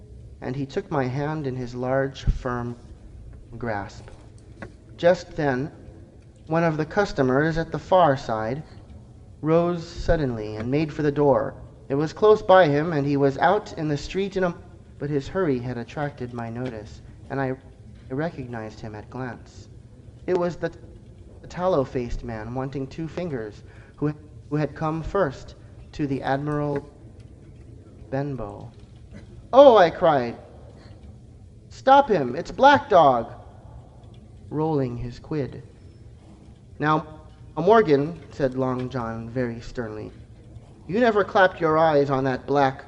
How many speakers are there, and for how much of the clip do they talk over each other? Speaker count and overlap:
1, no overlap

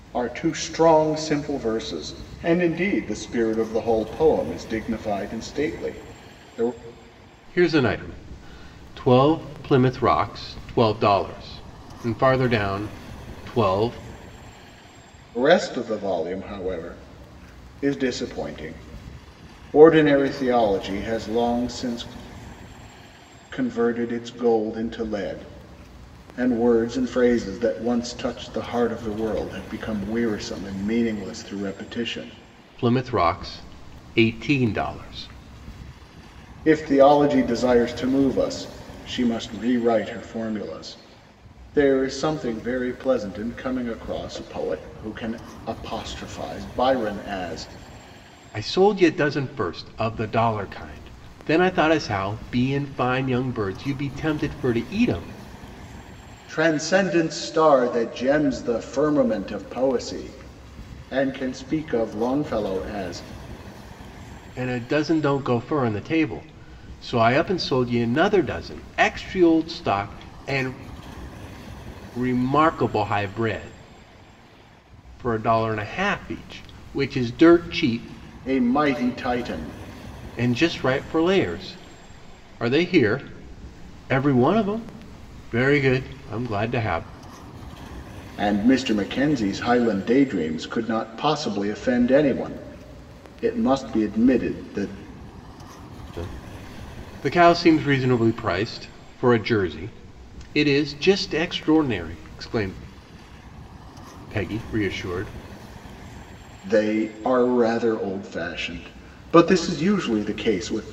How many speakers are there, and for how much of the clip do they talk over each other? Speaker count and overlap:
2, no overlap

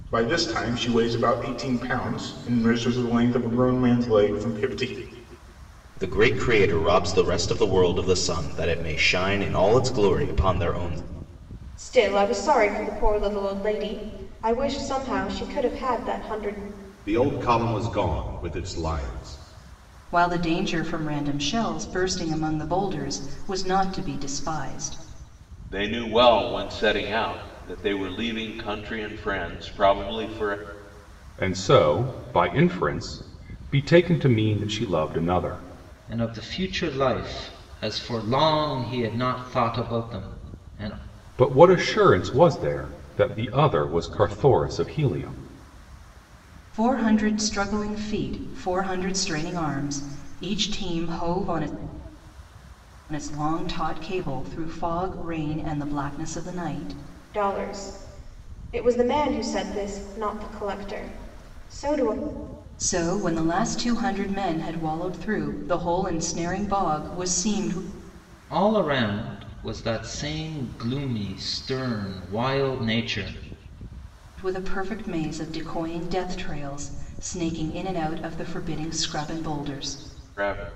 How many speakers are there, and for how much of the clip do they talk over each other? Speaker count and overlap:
8, no overlap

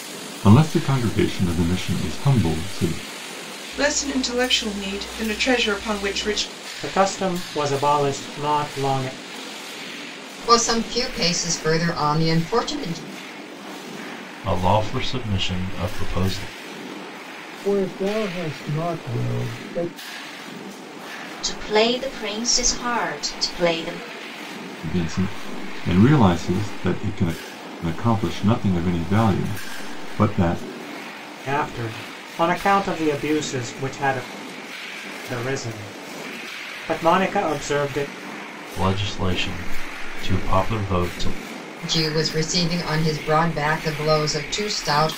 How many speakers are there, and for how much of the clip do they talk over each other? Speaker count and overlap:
7, no overlap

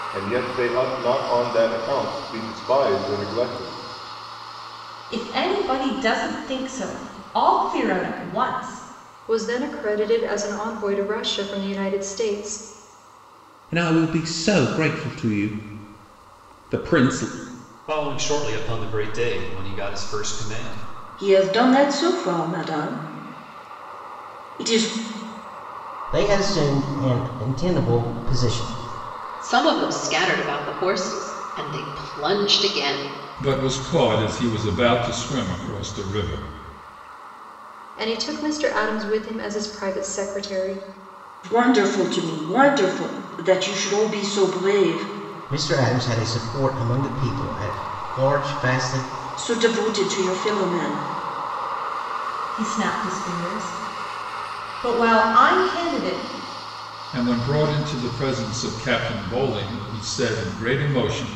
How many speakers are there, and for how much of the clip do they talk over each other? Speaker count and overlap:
9, no overlap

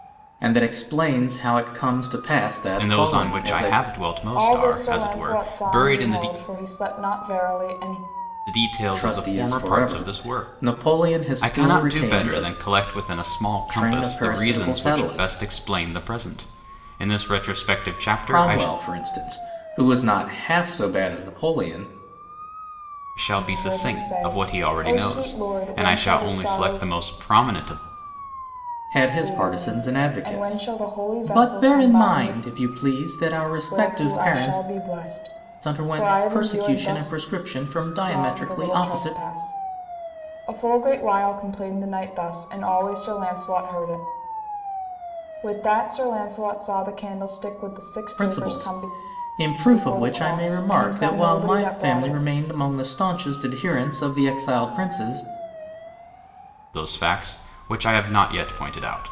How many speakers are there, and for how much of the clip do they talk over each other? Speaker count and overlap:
3, about 36%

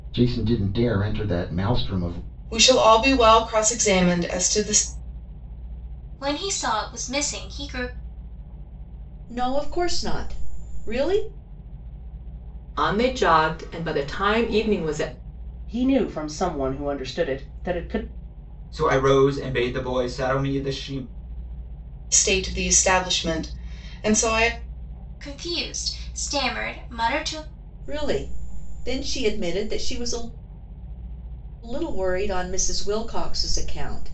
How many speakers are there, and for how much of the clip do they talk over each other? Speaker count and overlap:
7, no overlap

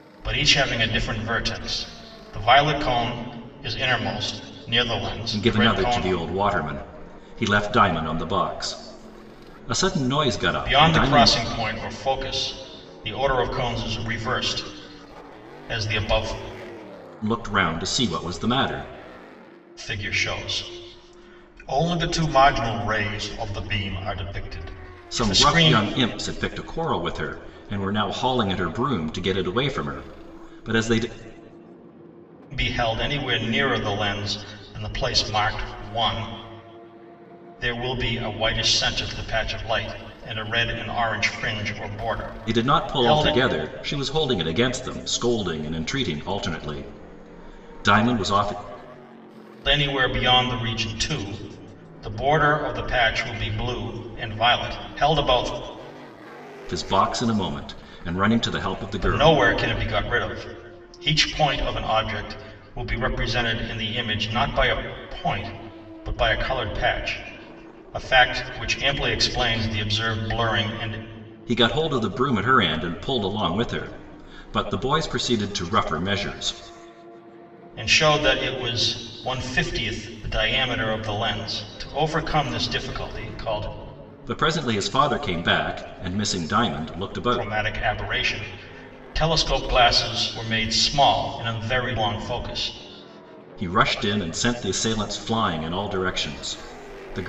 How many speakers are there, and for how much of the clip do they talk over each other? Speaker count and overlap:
2, about 4%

